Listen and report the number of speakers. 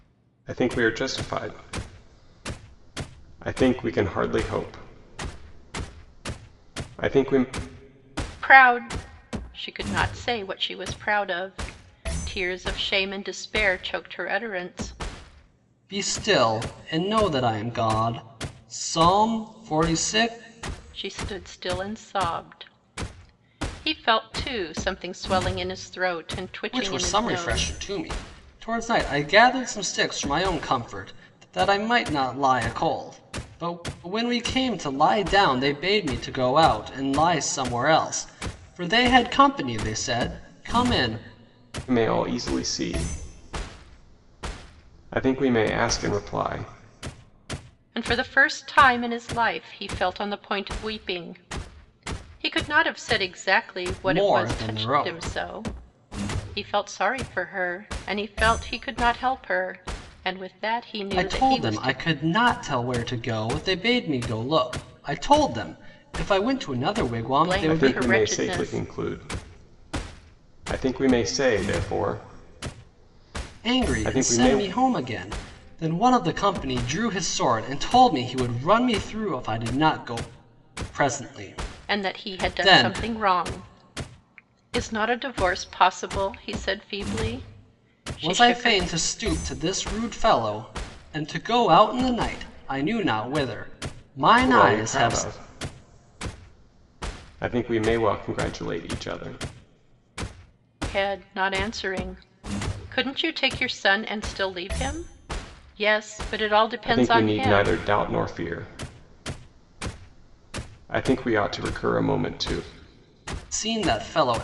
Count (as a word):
three